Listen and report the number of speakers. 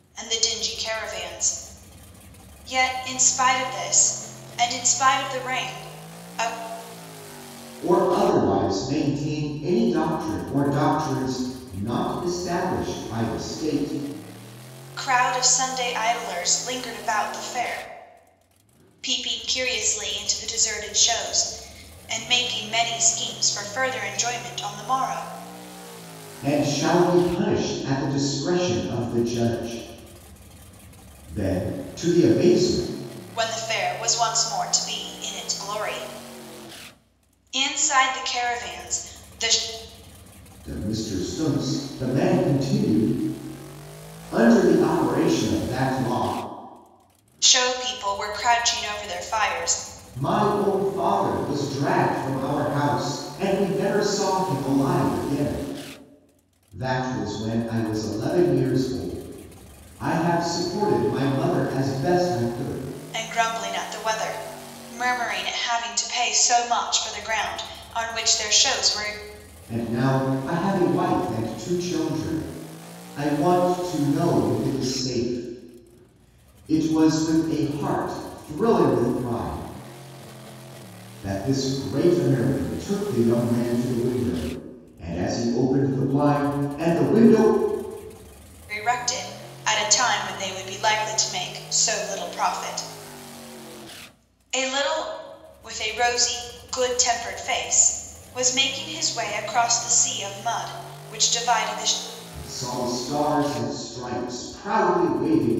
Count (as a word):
two